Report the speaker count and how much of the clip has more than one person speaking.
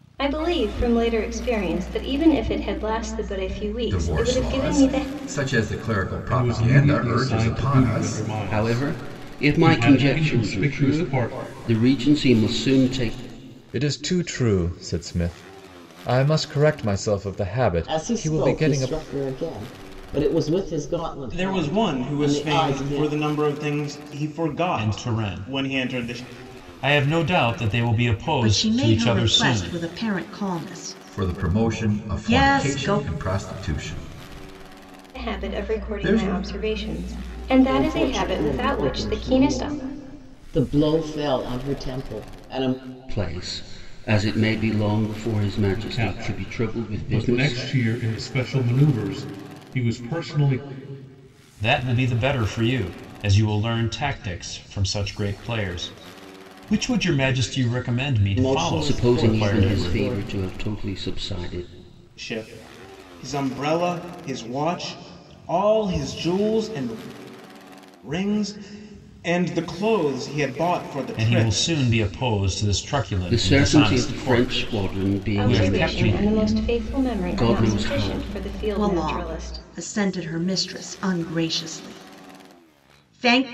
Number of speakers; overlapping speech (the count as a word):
nine, about 33%